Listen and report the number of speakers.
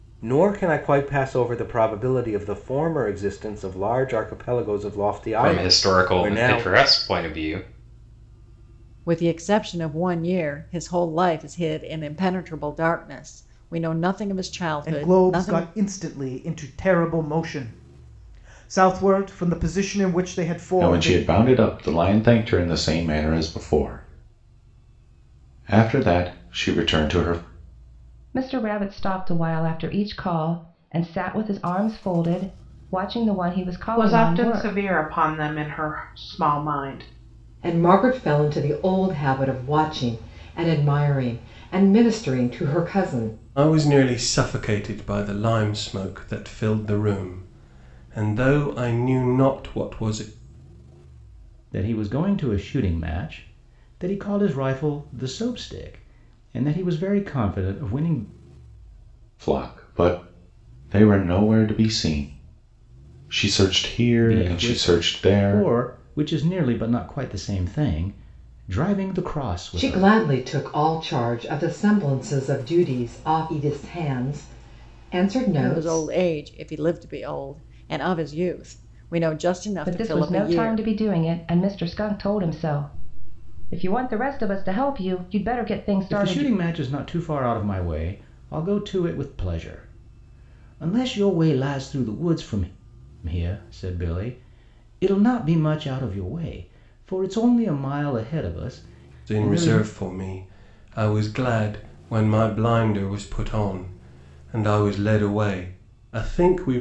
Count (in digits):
10